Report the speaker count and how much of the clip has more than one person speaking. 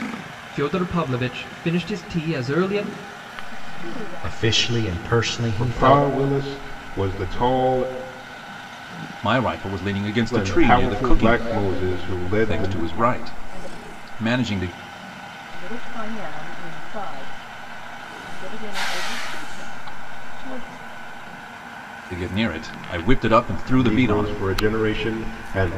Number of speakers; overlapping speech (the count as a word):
five, about 21%